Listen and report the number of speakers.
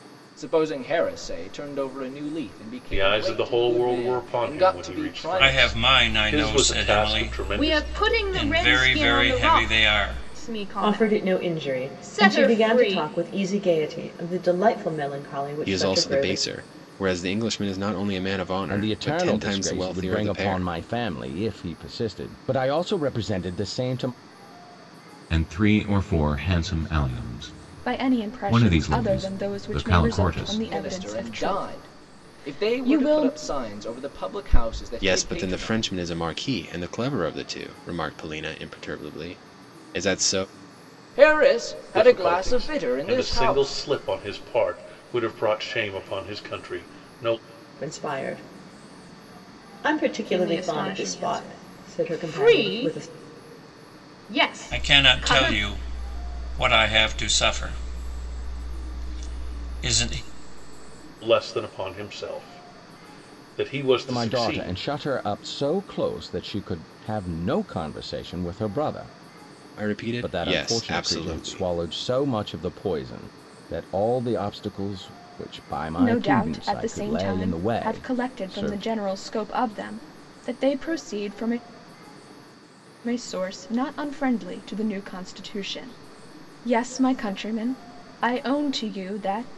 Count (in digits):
9